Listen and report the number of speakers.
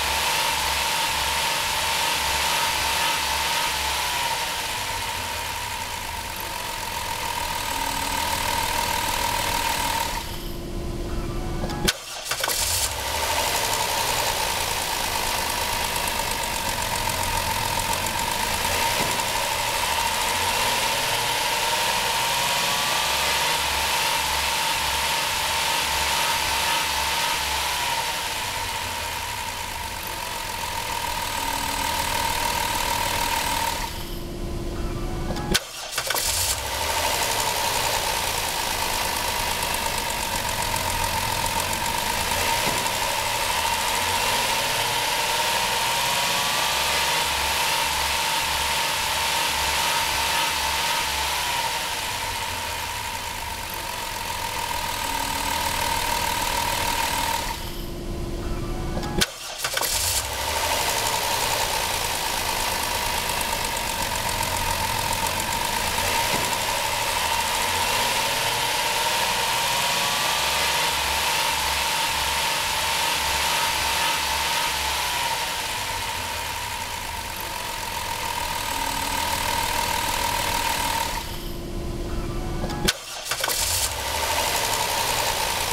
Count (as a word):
zero